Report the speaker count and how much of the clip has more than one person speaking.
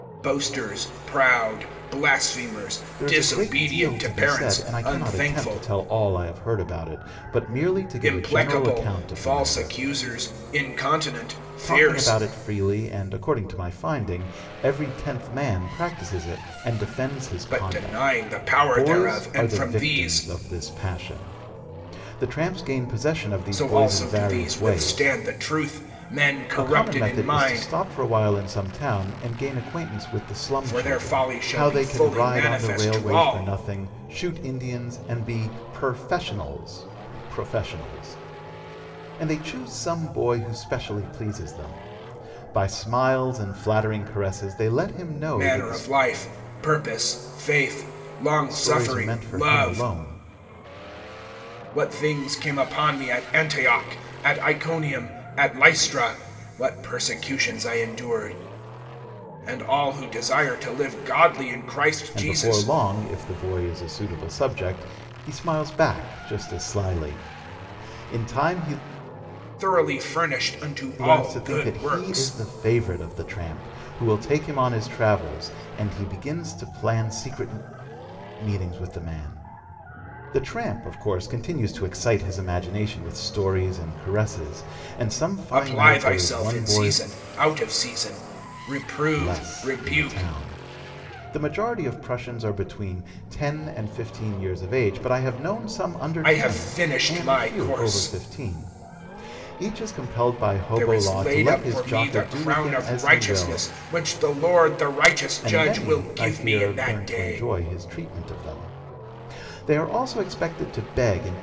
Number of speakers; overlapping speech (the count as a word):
two, about 24%